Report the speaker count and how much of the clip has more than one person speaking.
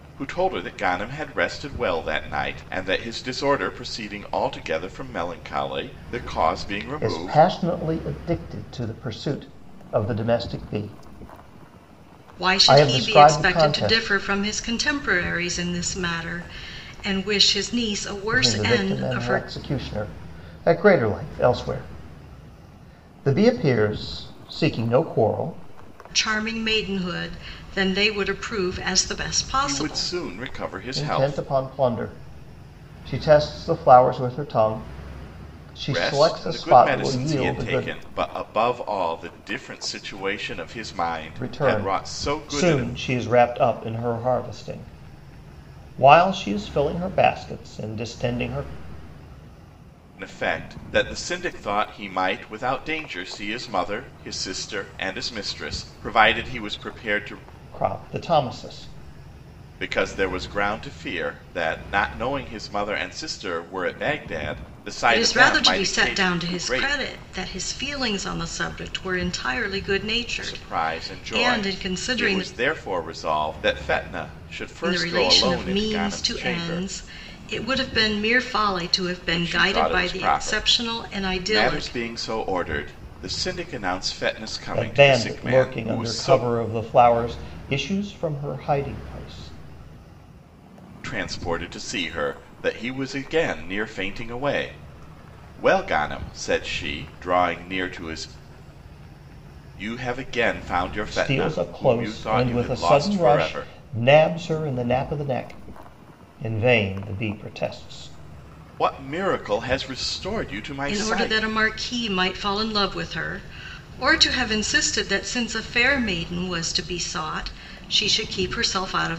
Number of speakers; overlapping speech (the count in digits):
3, about 19%